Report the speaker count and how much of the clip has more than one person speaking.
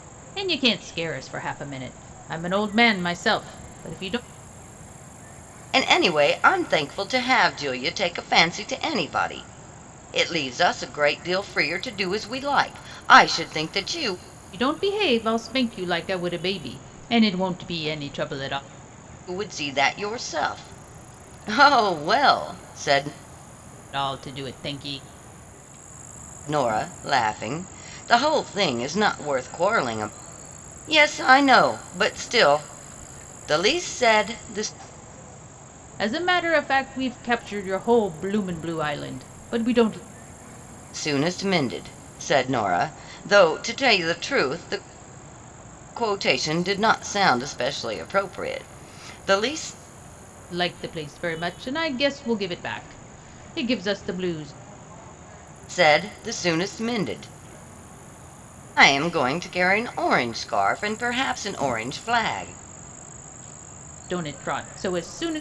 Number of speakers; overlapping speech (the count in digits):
2, no overlap